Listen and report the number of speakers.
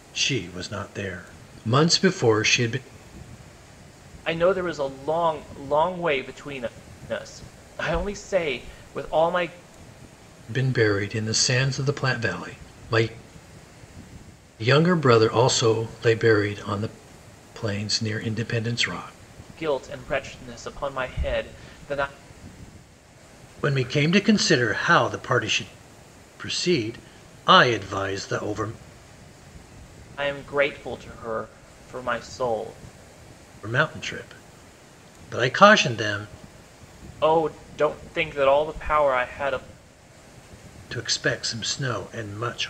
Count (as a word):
two